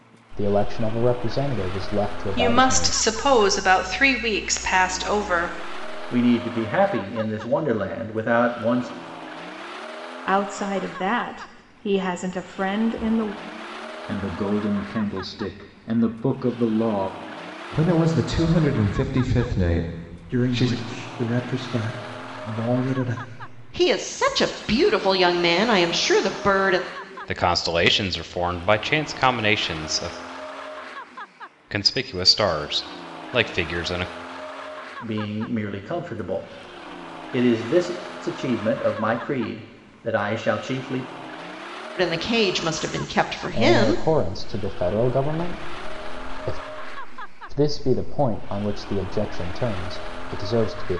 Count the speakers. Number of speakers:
9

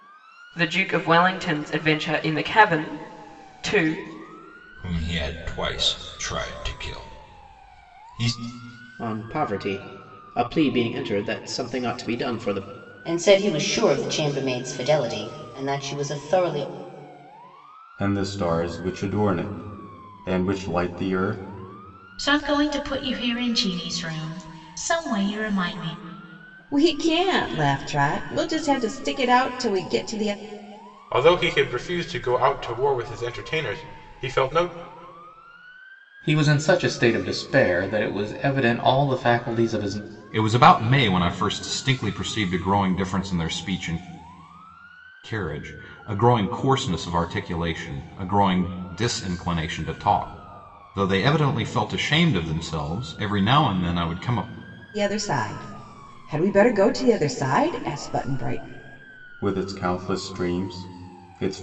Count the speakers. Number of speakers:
10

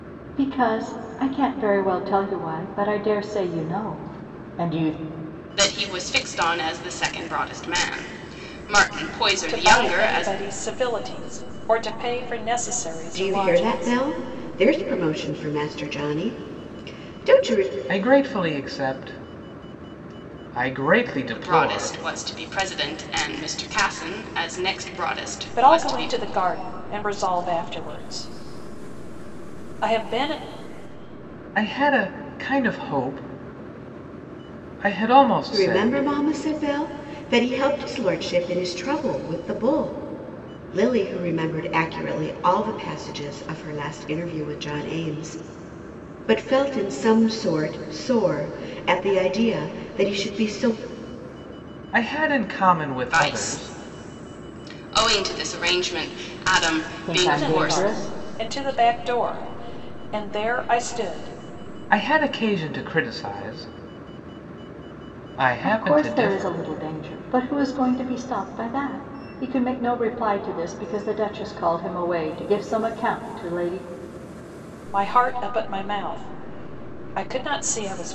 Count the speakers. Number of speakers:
5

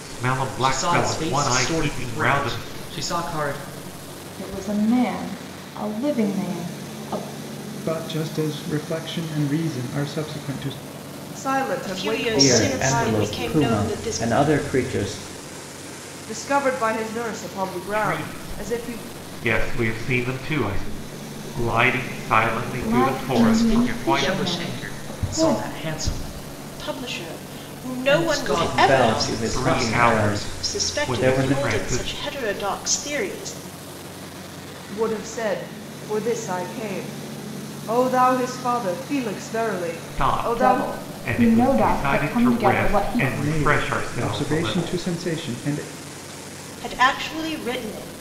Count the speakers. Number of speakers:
7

